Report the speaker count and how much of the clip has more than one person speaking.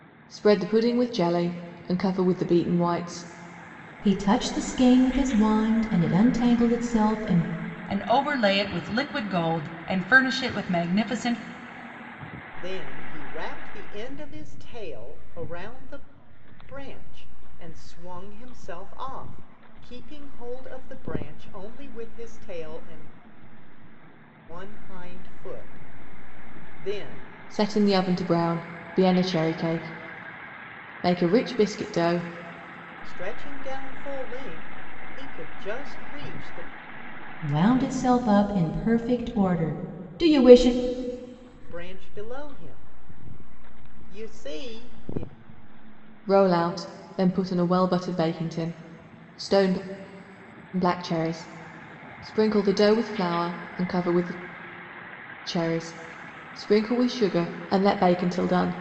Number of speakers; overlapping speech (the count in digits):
4, no overlap